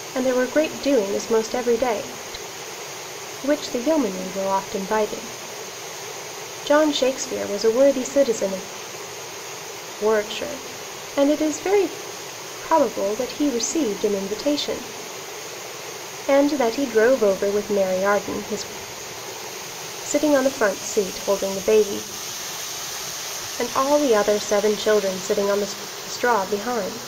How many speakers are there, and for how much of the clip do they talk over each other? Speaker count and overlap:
1, no overlap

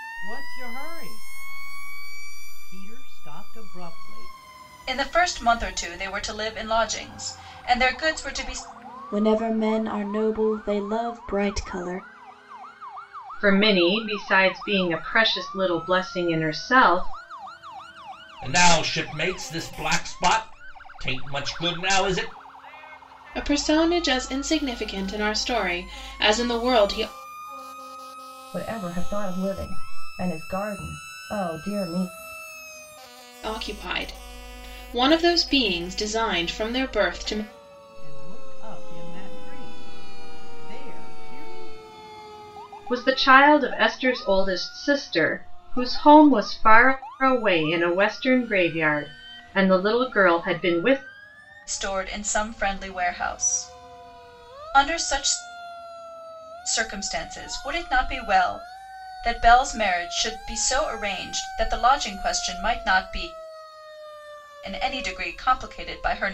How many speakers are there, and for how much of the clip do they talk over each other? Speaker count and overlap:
7, no overlap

